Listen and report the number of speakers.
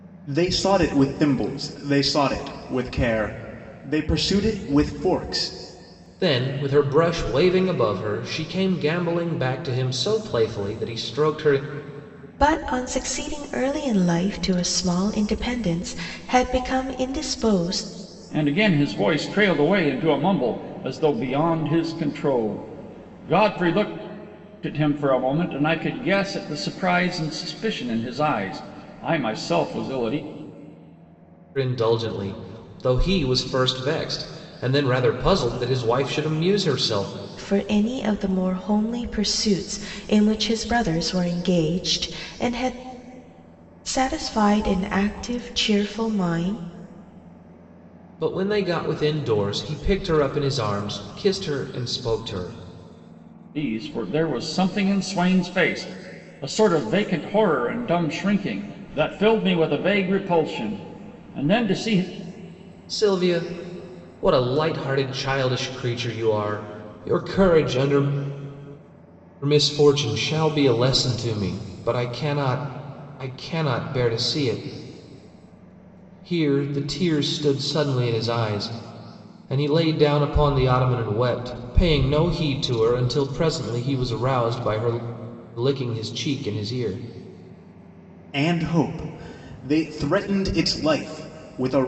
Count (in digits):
4